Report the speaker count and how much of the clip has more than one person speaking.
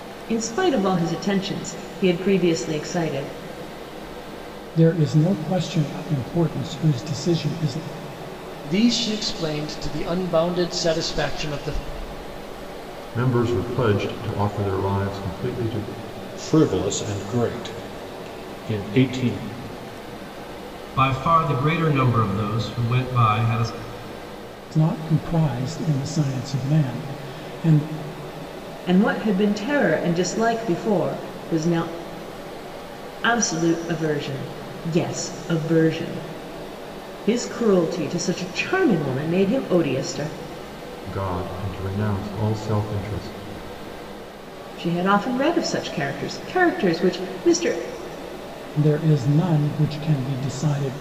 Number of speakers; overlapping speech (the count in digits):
6, no overlap